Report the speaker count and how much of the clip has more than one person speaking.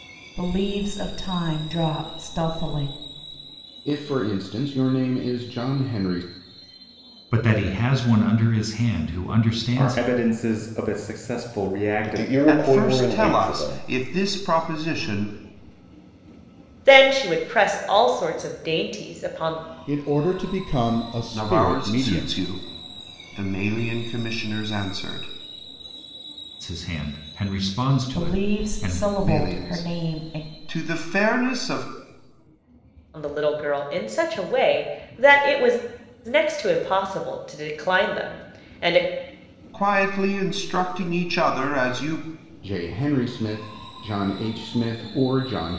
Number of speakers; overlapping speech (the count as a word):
eight, about 12%